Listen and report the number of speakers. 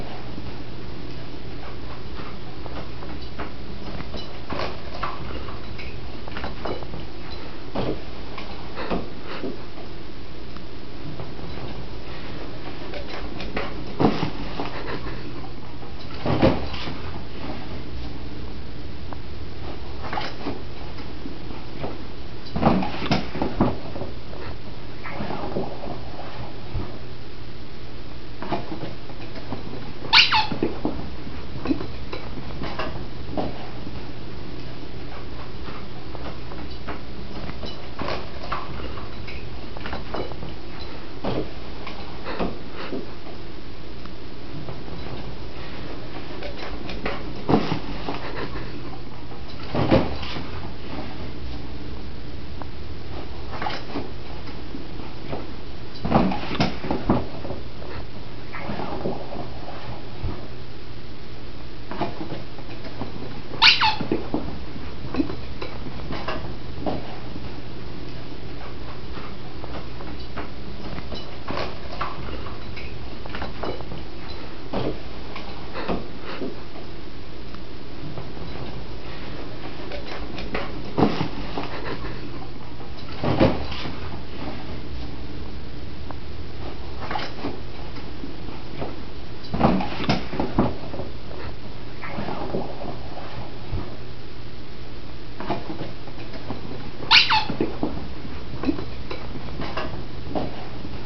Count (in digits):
0